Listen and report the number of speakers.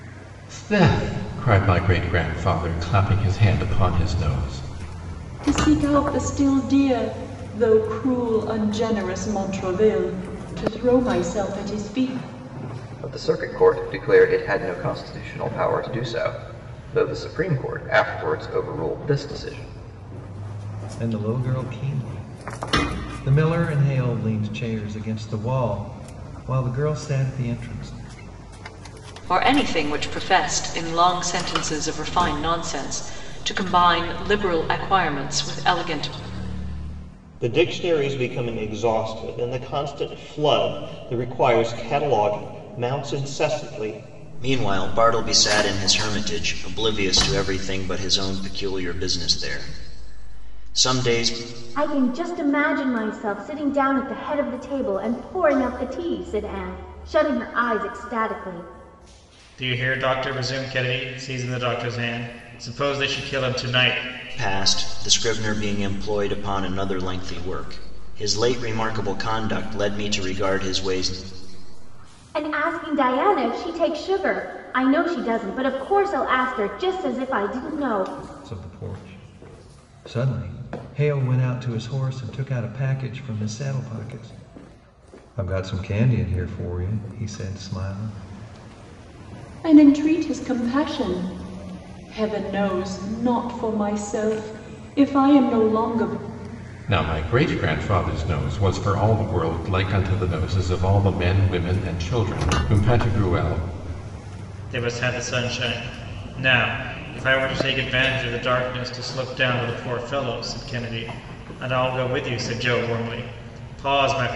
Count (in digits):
9